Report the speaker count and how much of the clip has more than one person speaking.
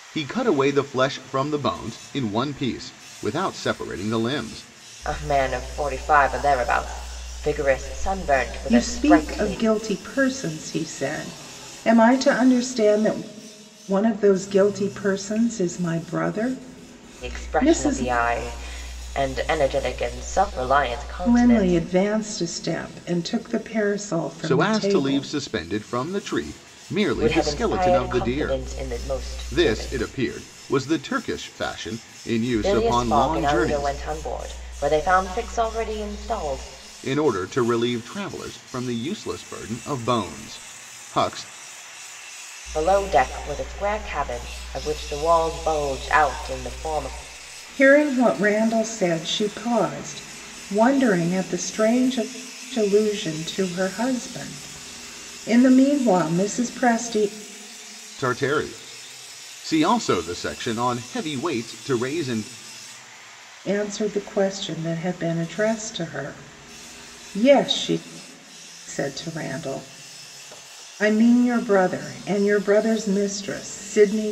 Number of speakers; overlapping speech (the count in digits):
3, about 9%